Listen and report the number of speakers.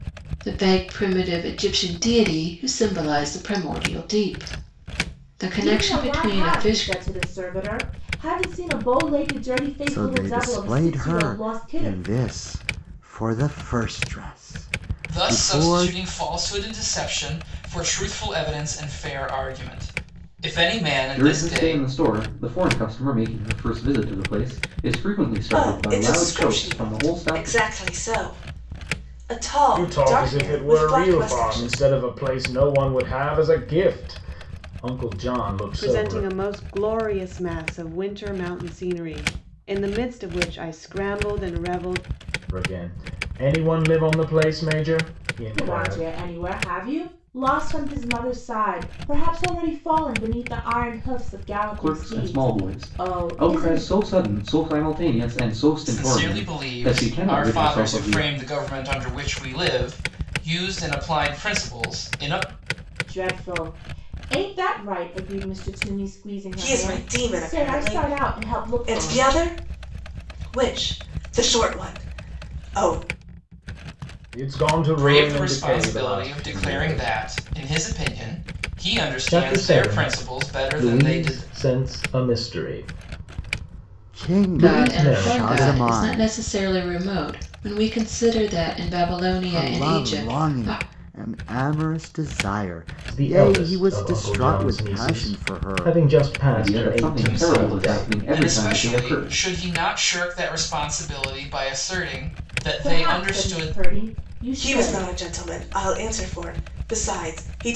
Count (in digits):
8